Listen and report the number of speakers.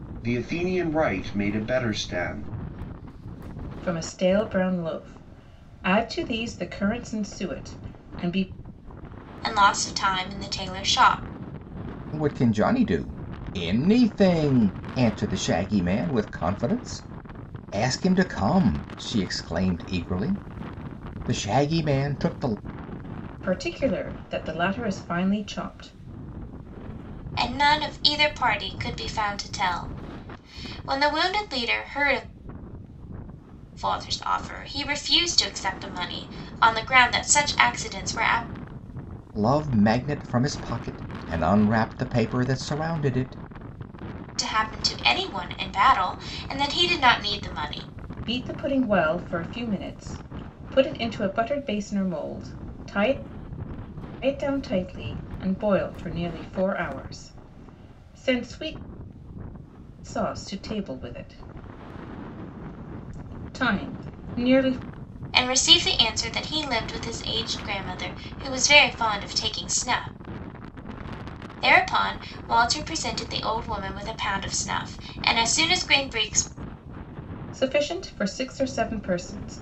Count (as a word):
four